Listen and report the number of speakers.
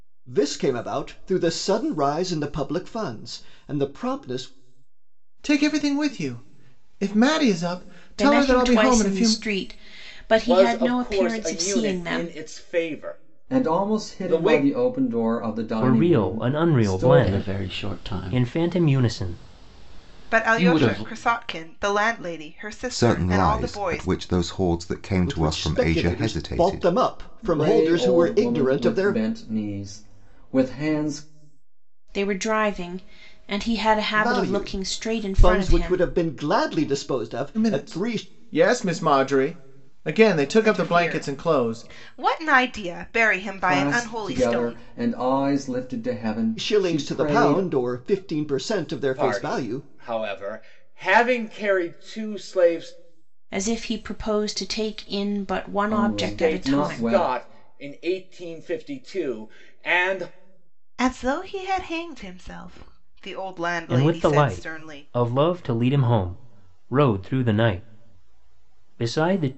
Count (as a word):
nine